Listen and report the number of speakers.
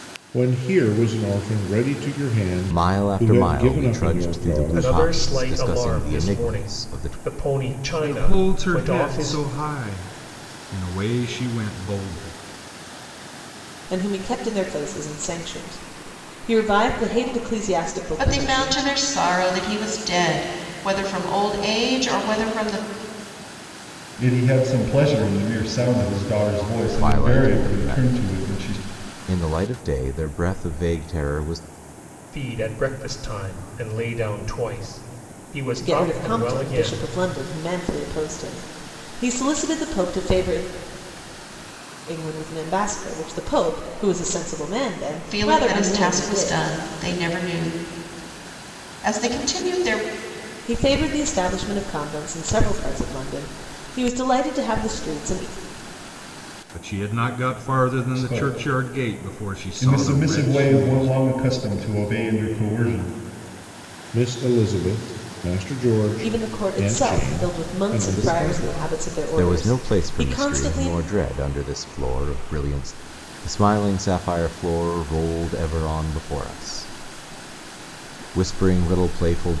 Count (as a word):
seven